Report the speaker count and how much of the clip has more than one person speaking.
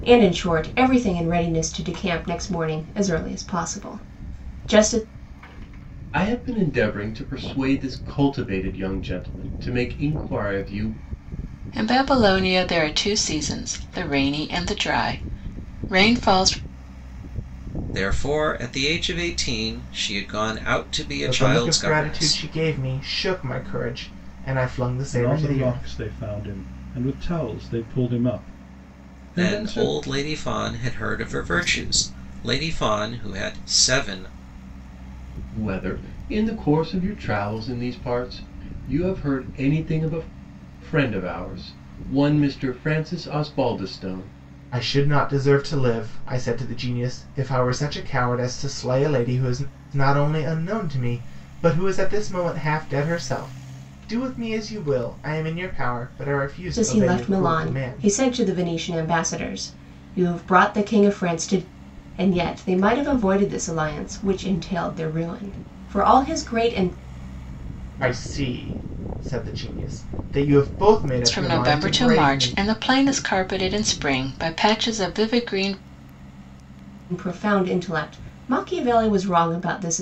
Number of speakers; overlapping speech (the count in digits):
6, about 7%